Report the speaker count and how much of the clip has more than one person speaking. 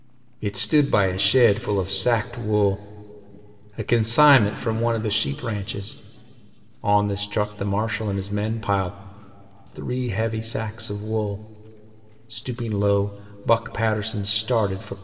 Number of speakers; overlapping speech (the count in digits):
1, no overlap